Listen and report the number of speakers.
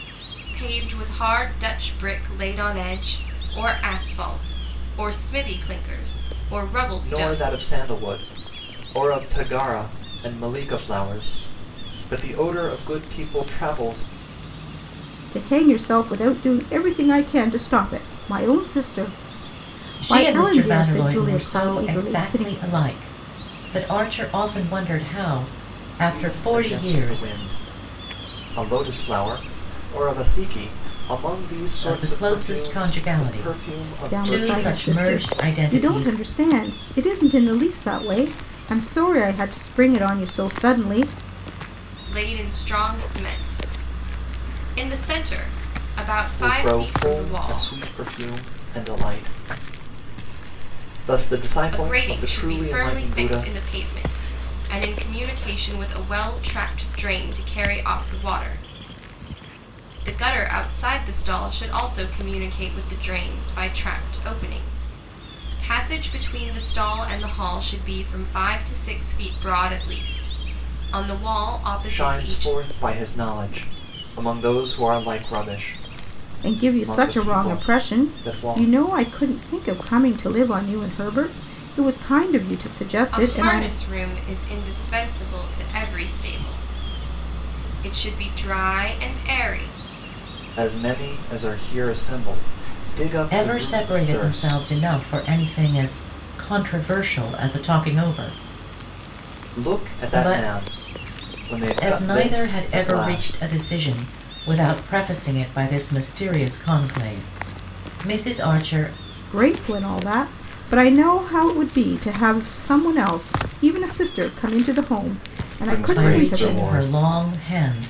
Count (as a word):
four